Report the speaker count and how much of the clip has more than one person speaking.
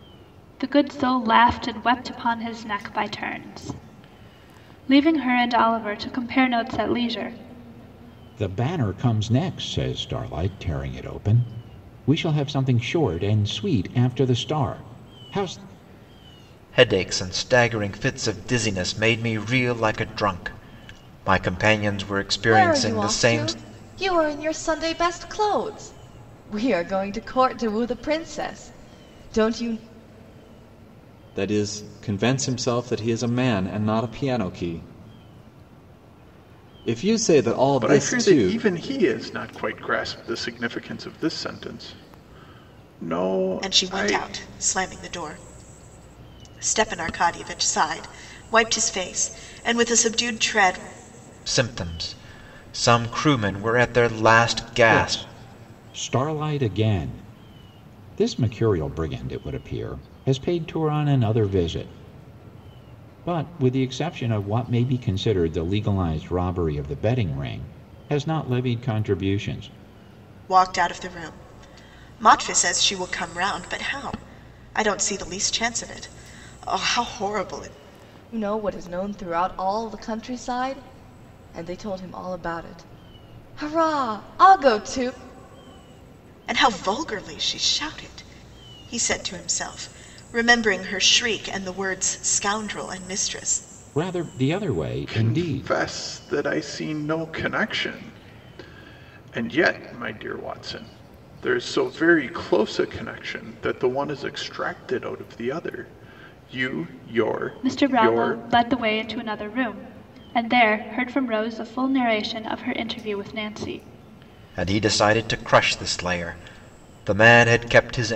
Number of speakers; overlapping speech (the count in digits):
7, about 4%